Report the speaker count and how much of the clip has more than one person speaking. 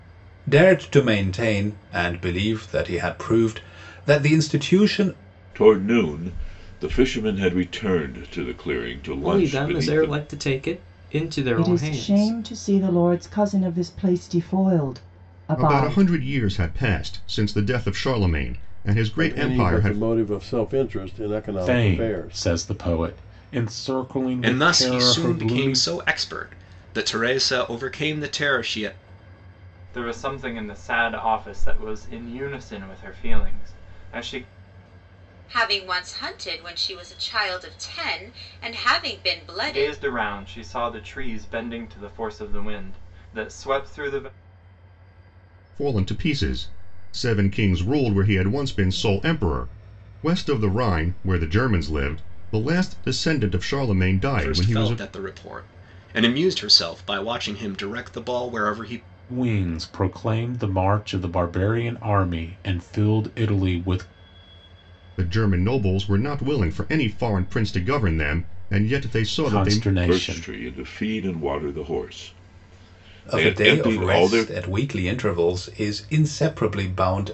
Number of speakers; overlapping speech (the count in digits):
10, about 11%